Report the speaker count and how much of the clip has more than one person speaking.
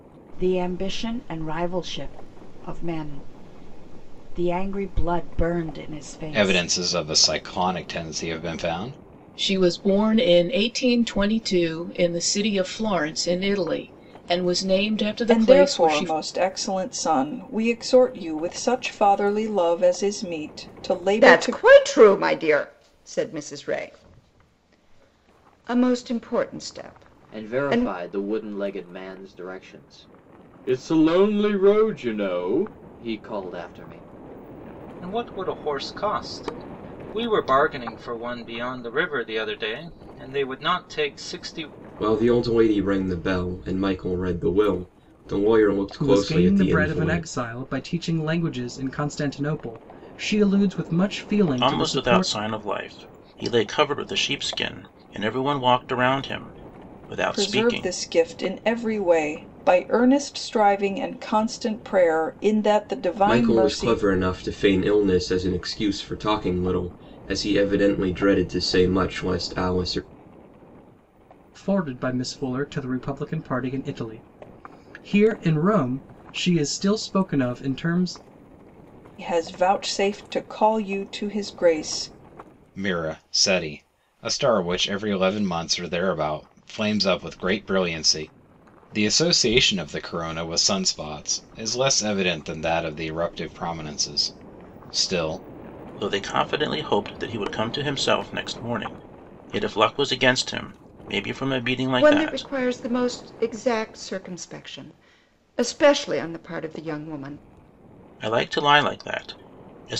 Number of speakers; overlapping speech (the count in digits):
10, about 6%